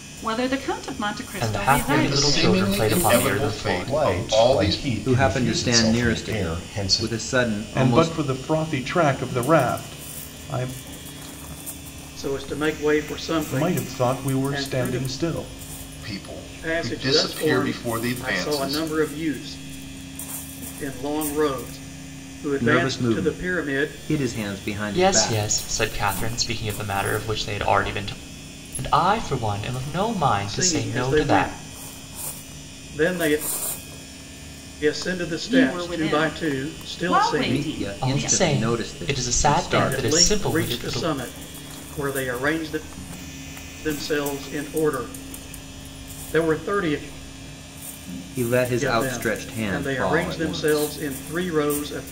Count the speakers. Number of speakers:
7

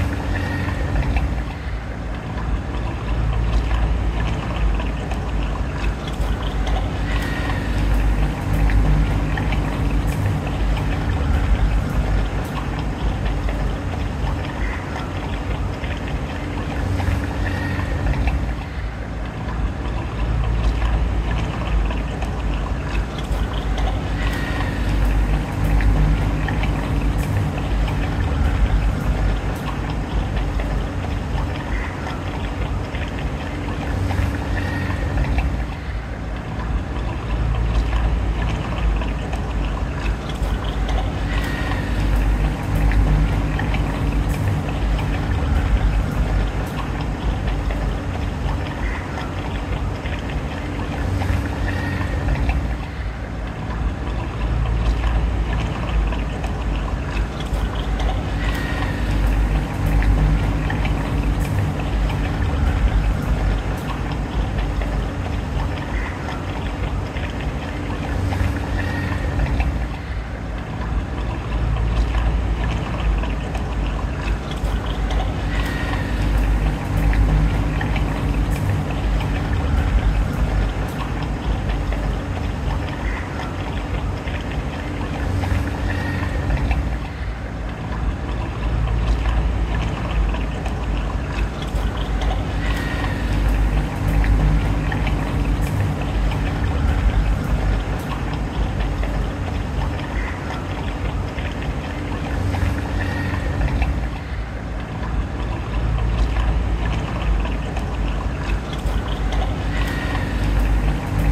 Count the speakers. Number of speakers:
0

